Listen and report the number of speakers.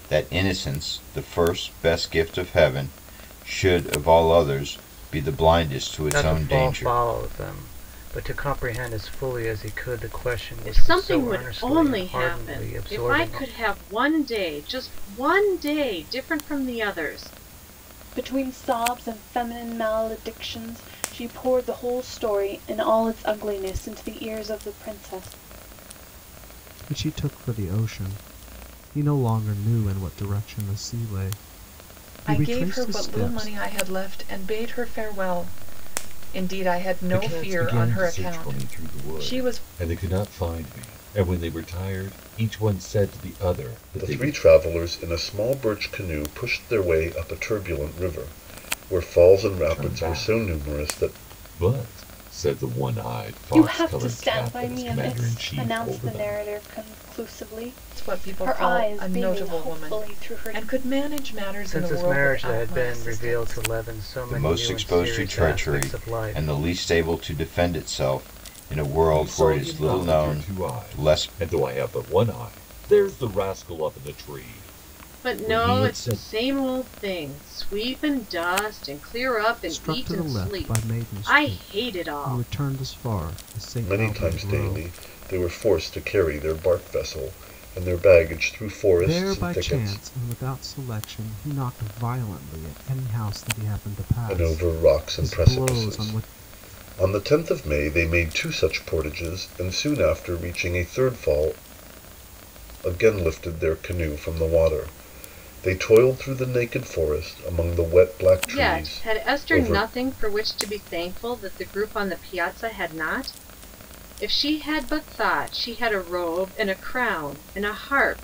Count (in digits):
8